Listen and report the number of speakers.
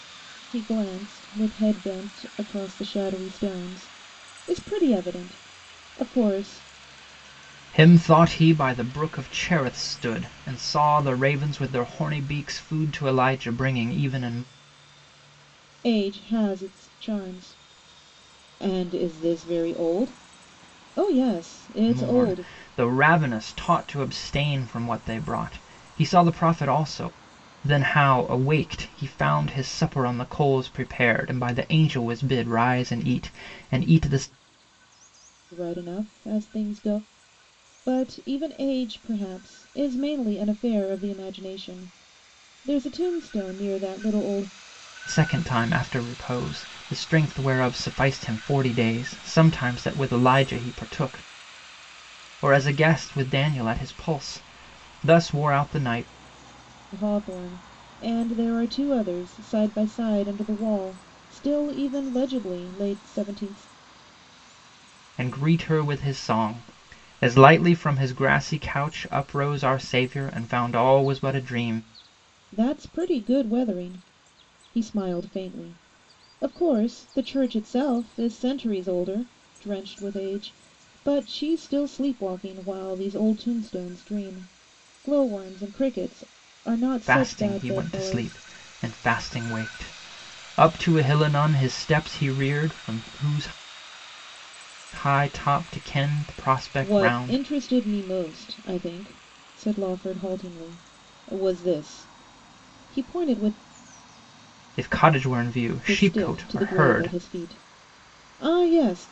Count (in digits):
2